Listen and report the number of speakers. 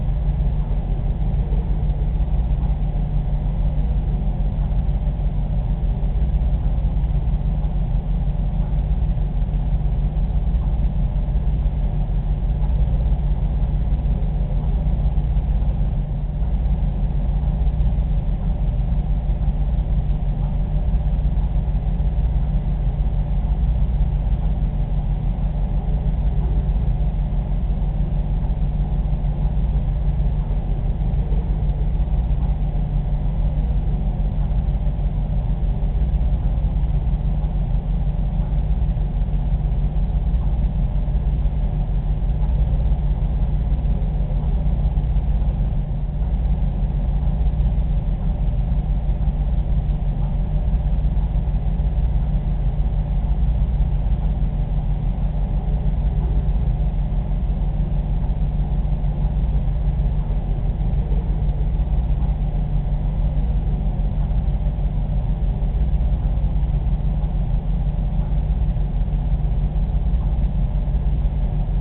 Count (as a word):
zero